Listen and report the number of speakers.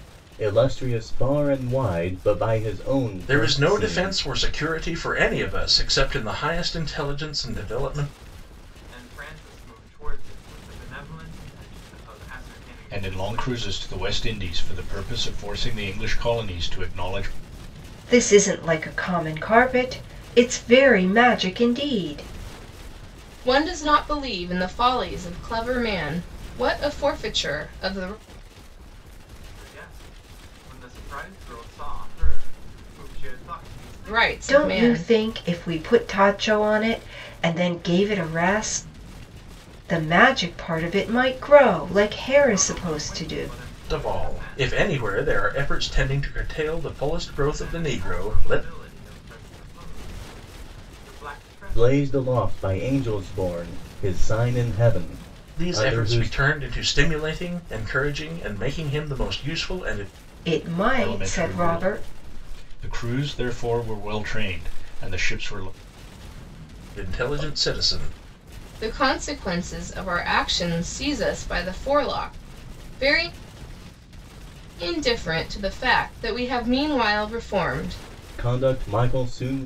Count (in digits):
6